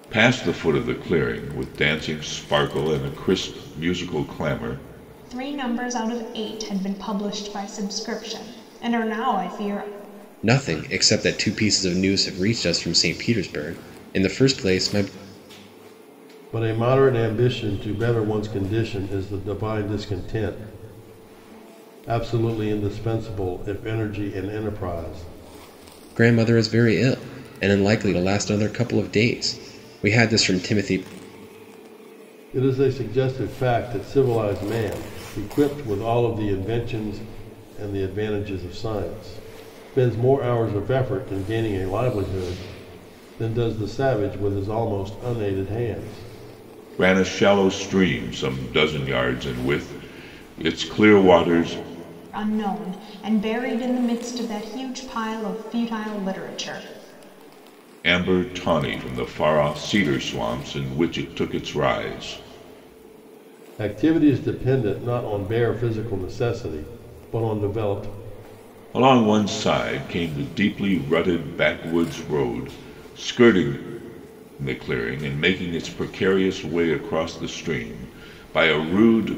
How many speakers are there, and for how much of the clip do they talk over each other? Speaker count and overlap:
four, no overlap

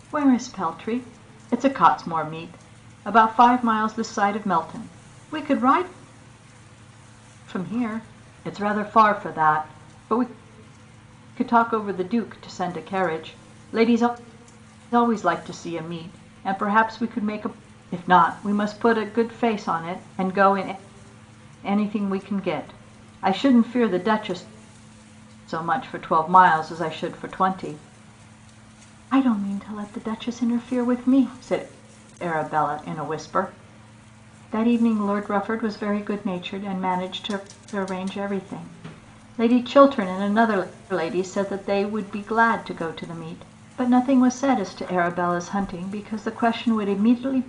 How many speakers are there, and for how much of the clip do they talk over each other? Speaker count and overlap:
one, no overlap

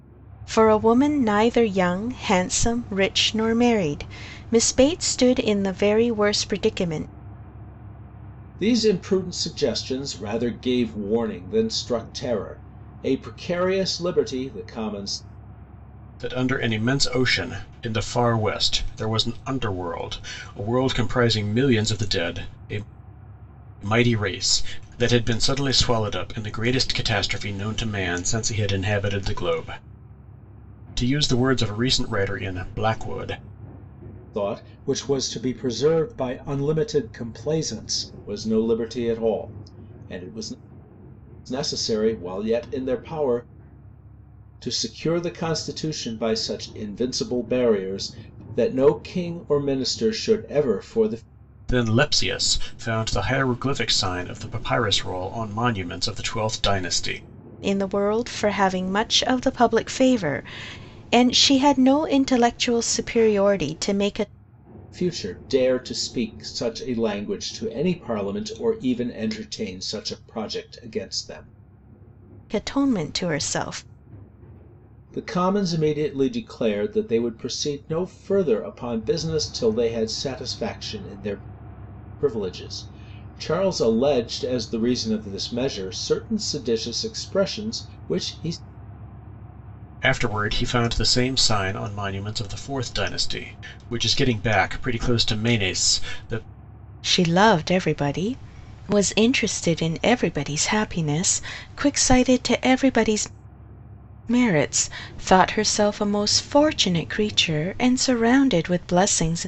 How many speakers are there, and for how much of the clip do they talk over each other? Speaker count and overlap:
three, no overlap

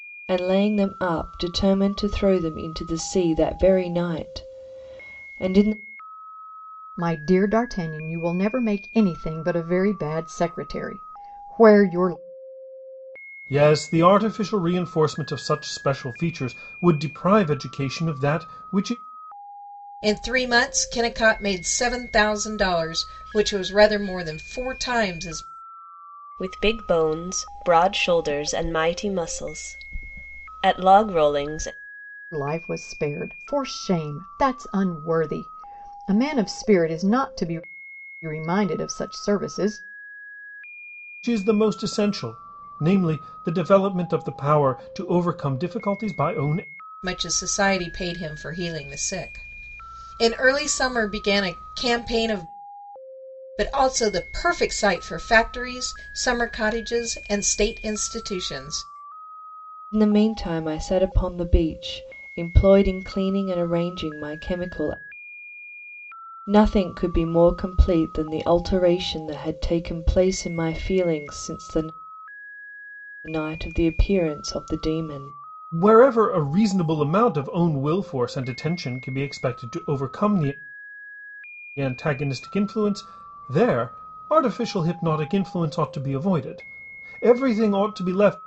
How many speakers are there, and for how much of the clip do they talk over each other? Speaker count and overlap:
five, no overlap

